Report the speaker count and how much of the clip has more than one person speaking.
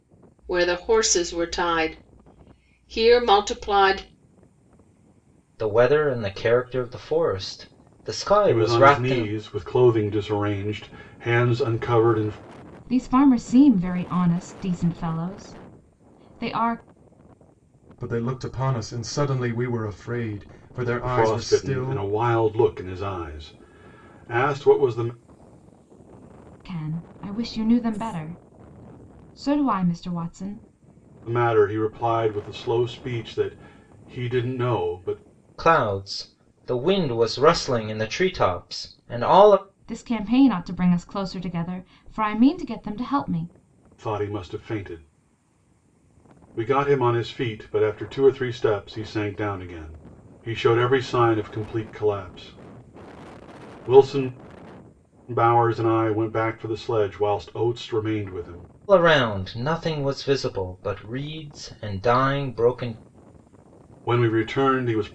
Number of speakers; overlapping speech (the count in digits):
5, about 3%